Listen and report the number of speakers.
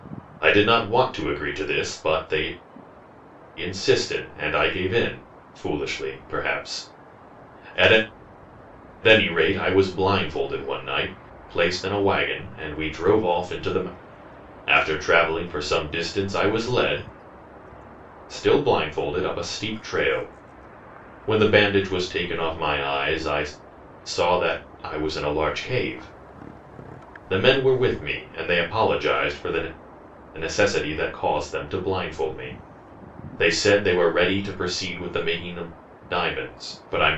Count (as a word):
one